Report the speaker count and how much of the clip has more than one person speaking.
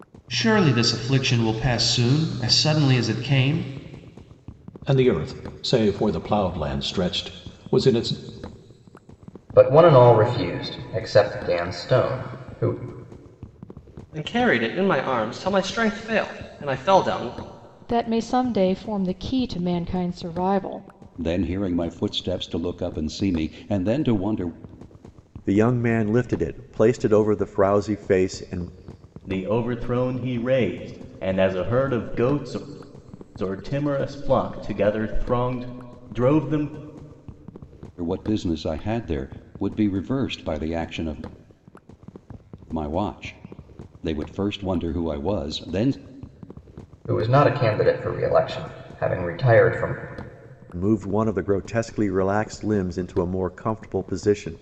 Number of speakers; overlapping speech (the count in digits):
8, no overlap